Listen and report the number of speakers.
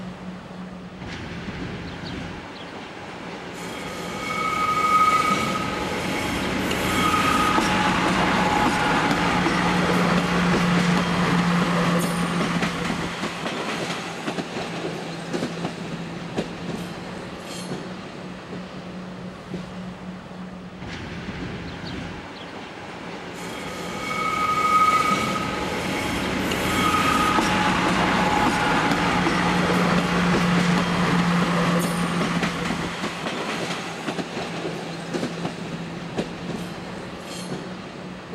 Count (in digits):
0